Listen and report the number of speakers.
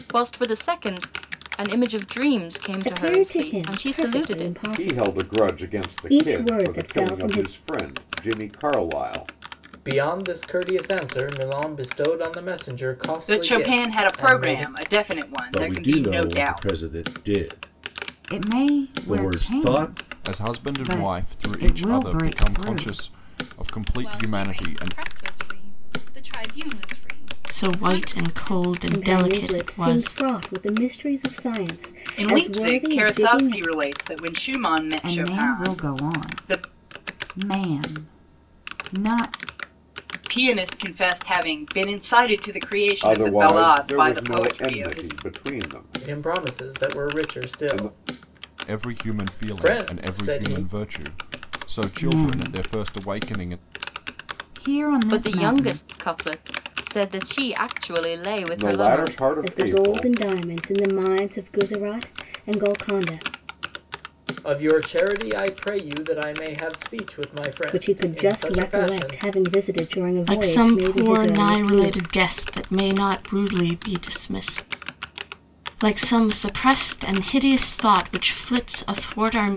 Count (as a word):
ten